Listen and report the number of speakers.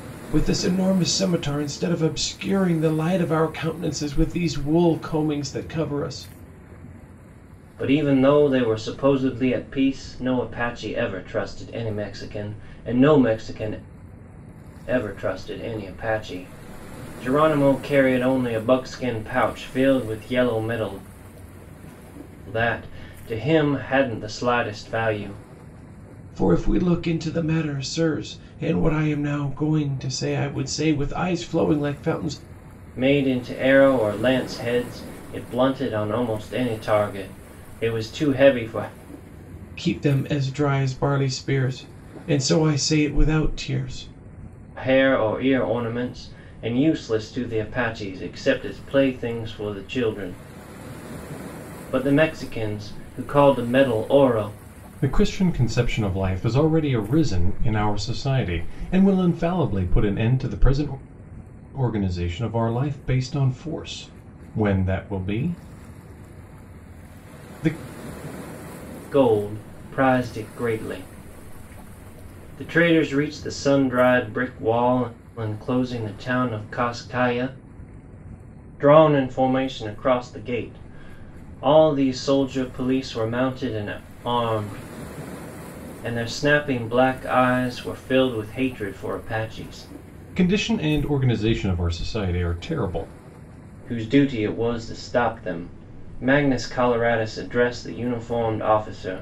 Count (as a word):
two